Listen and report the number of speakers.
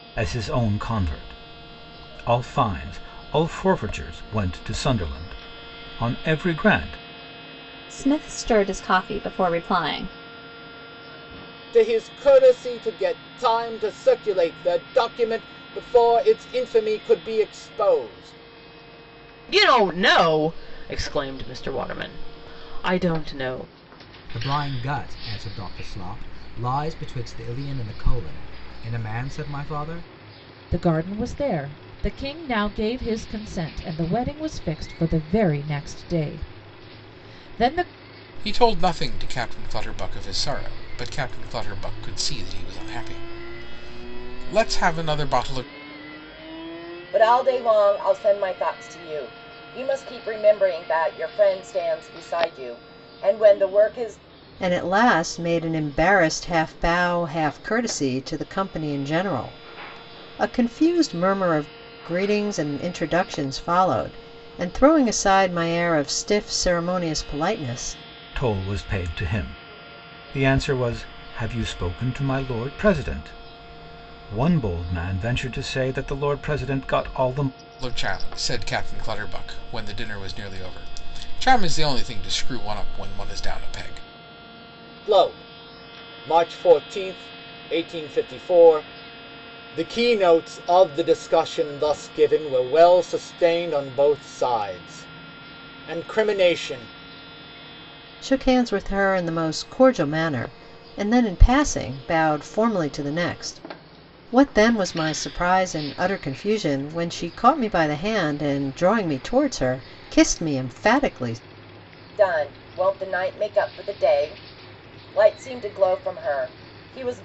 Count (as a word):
nine